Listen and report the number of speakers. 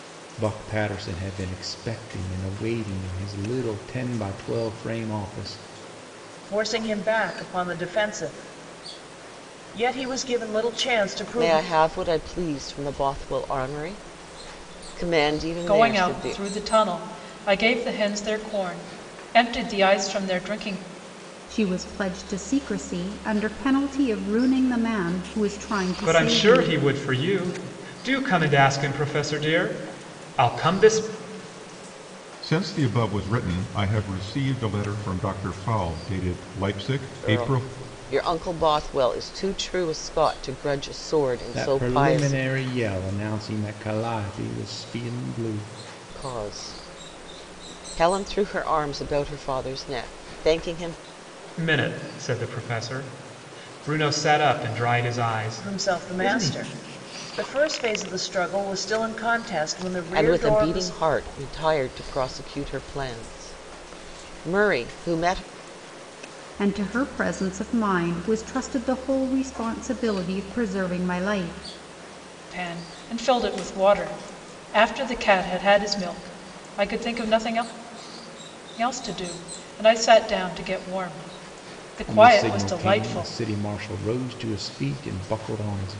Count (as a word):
seven